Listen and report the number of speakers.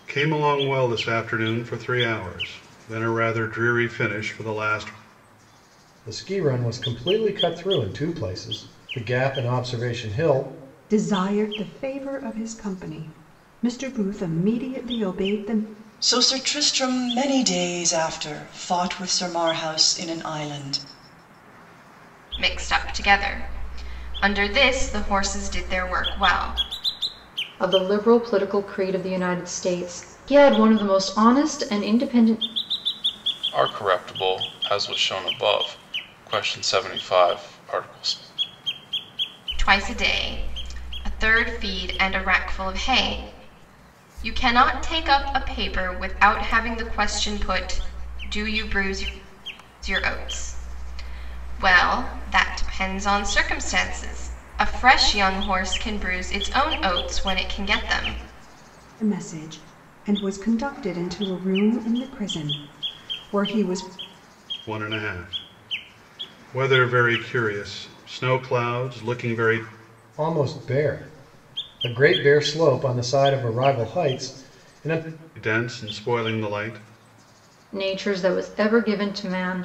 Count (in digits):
7